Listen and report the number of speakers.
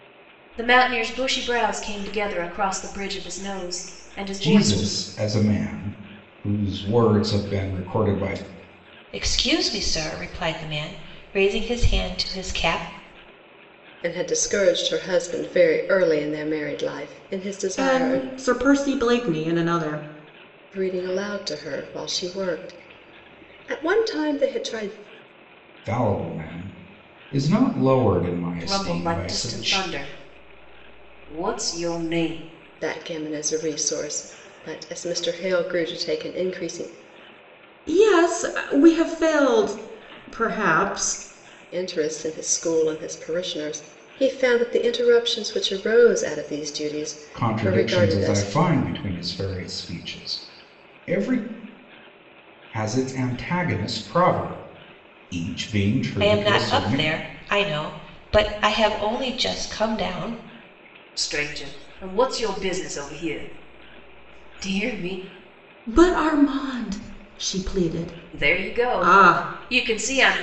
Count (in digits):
5